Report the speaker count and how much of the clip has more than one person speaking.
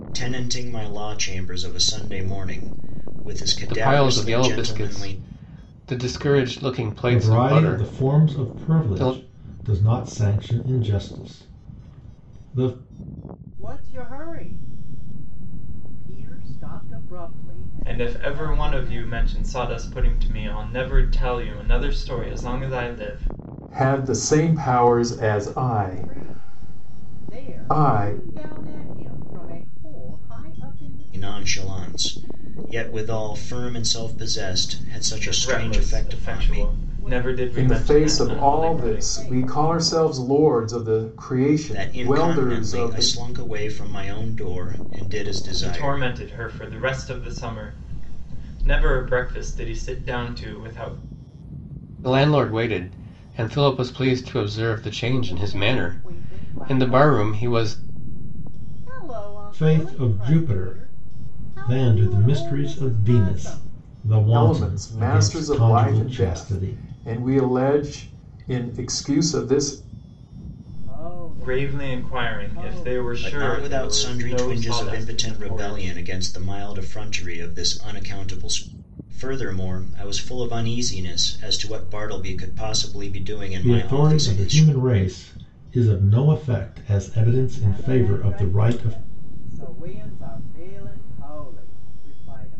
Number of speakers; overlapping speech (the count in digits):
6, about 33%